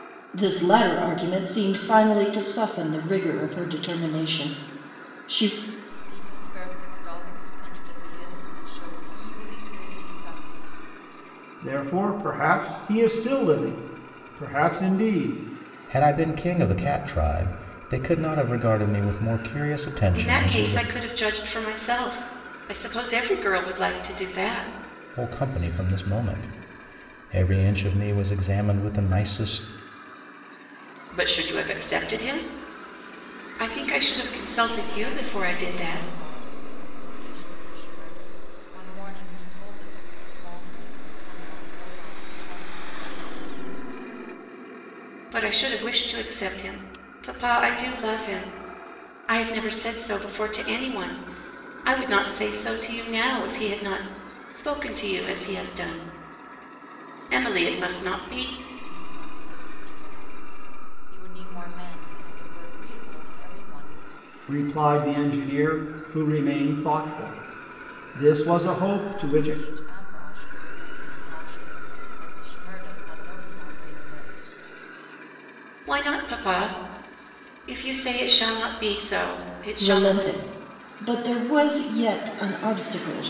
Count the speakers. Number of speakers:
five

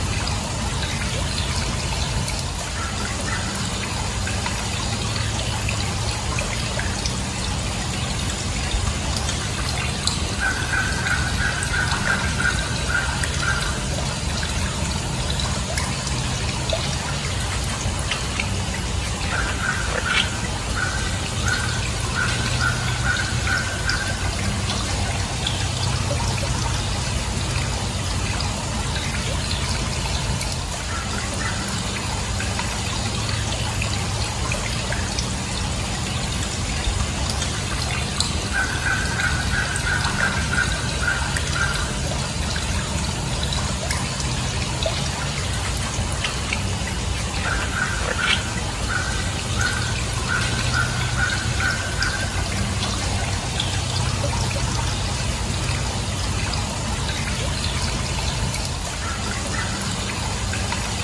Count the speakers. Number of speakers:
zero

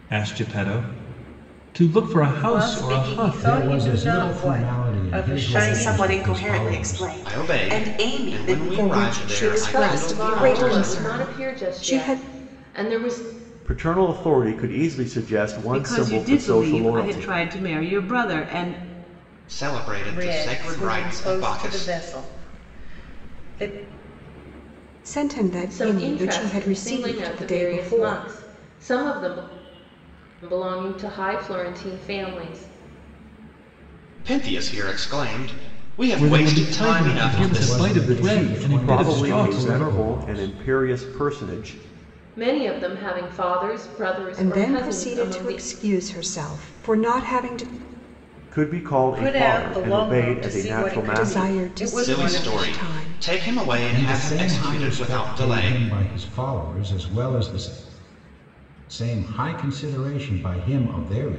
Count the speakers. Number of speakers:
nine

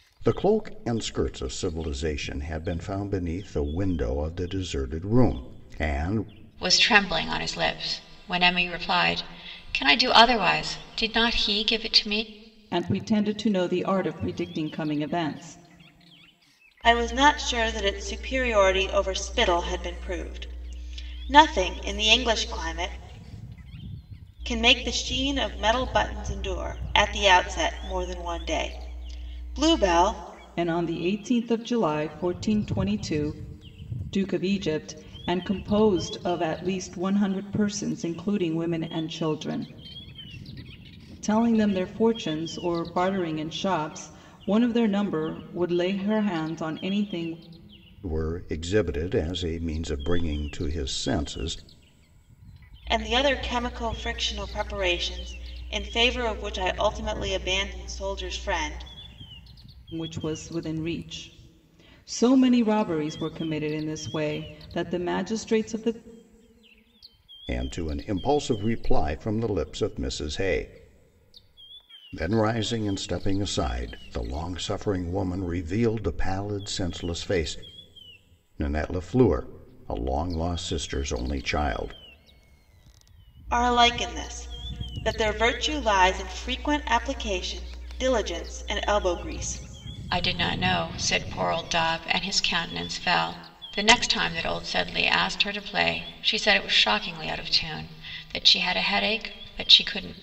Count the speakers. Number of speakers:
four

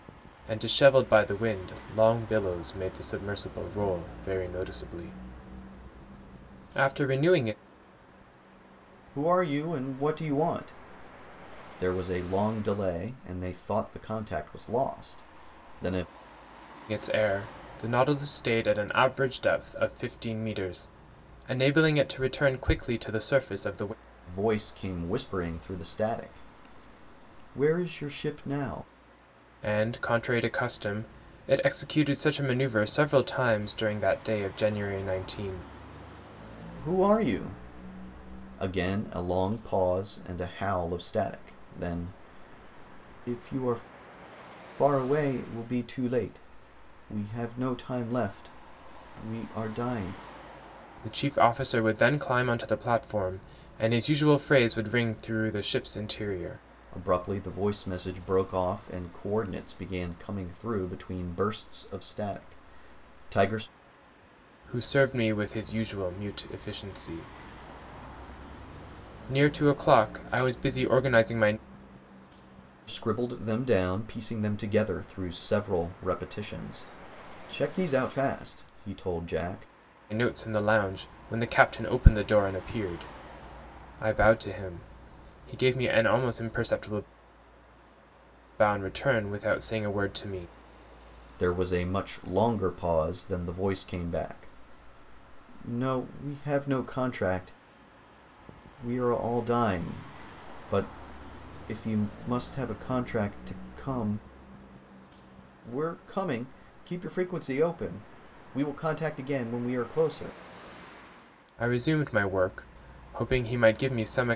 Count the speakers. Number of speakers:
two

